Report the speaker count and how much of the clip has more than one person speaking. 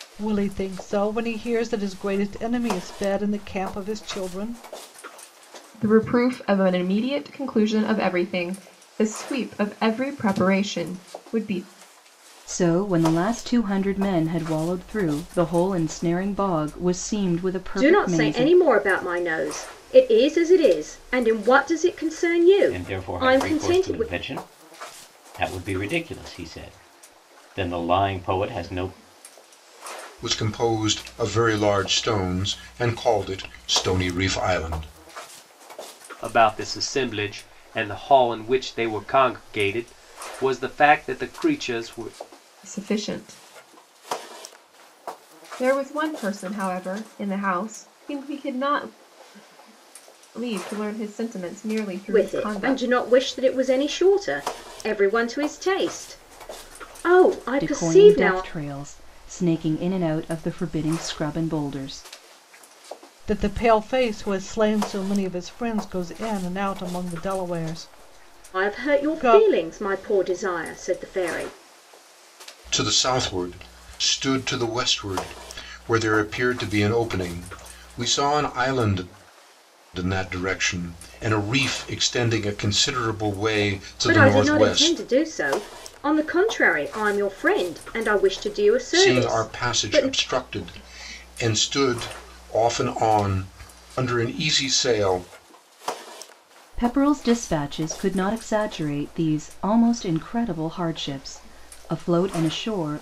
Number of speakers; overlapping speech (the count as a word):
seven, about 7%